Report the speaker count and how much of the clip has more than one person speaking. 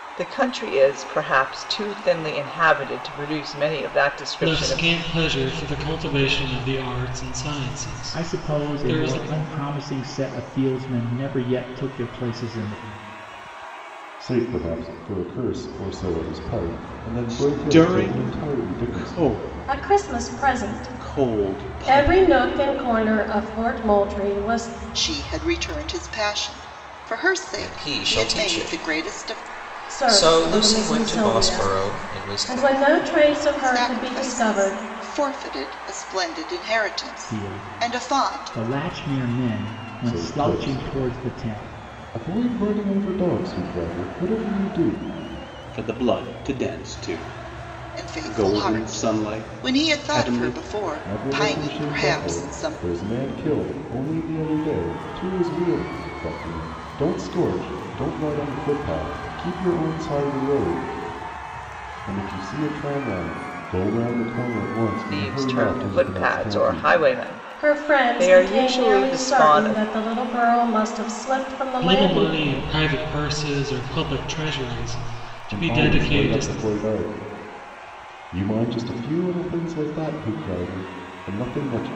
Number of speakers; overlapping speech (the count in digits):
8, about 31%